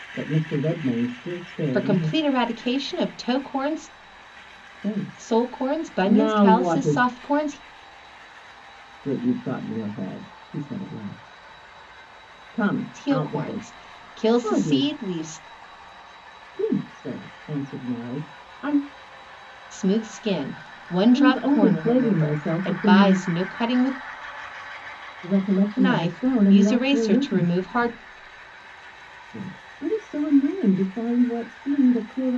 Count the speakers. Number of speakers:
2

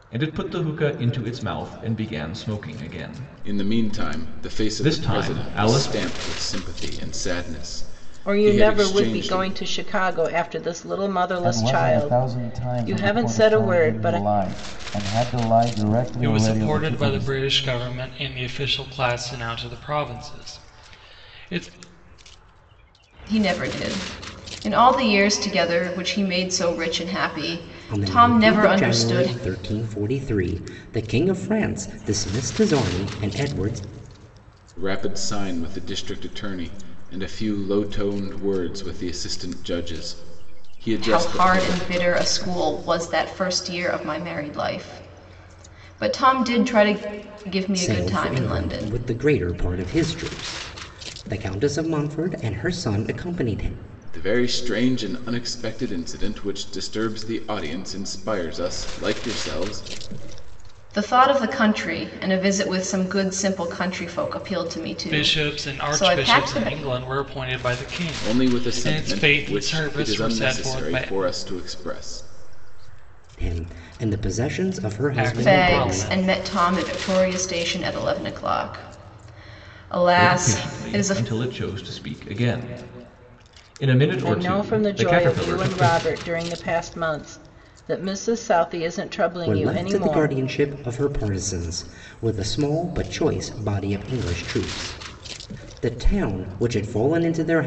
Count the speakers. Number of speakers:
7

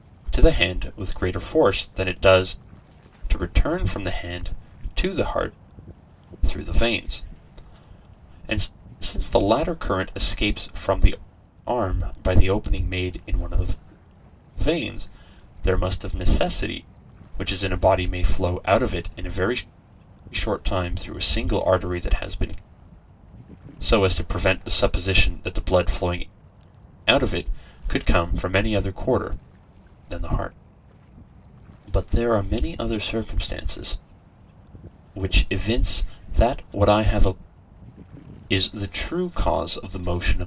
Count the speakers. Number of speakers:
1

